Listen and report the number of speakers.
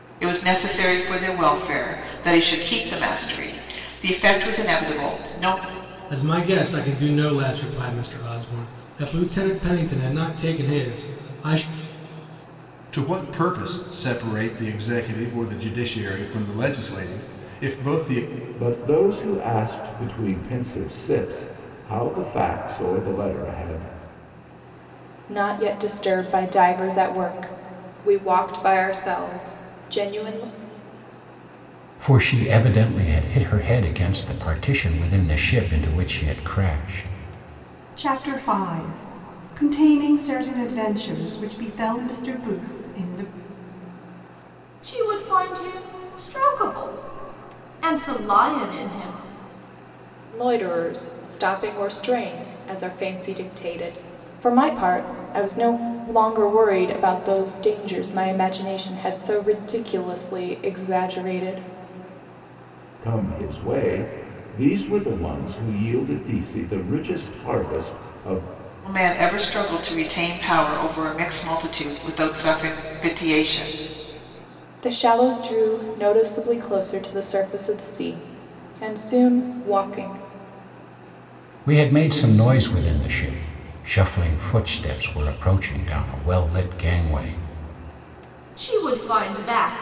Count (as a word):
eight